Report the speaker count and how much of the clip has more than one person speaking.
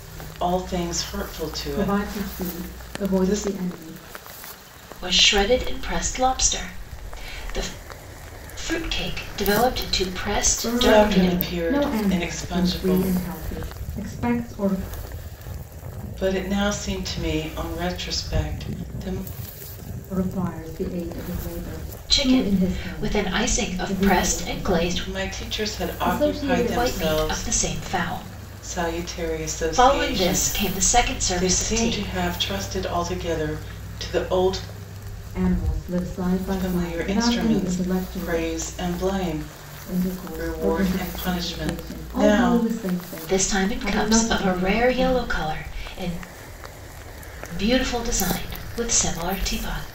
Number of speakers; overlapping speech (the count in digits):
3, about 36%